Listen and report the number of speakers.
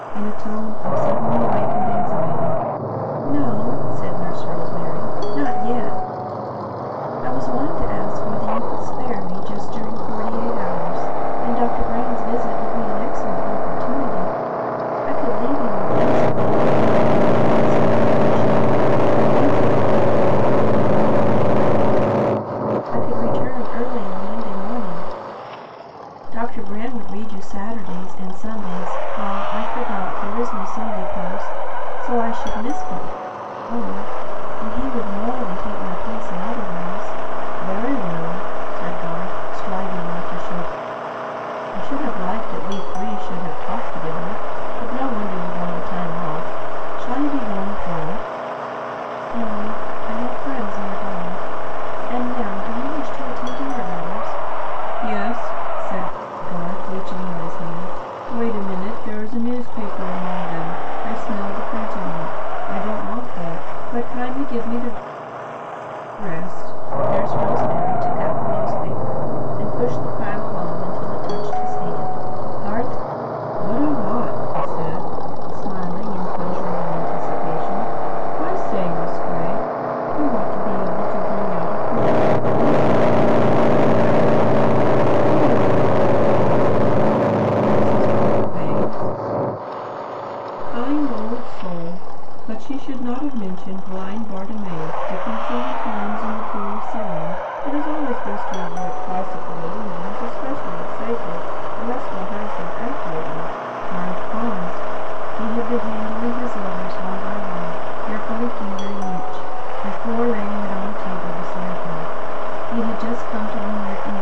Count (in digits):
1